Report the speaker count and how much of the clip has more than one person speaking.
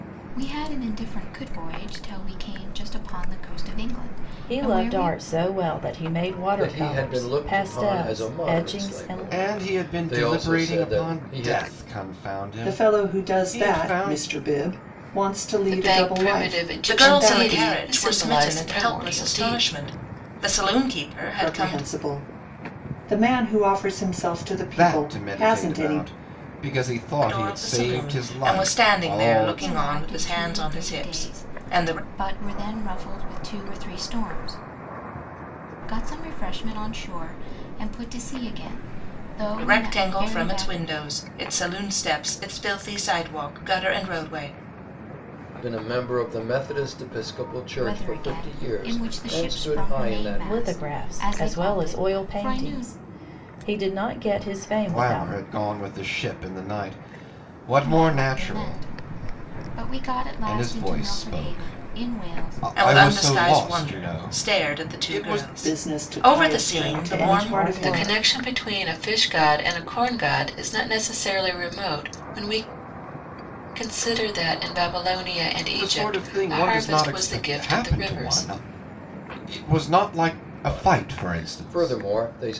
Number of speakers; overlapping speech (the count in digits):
7, about 47%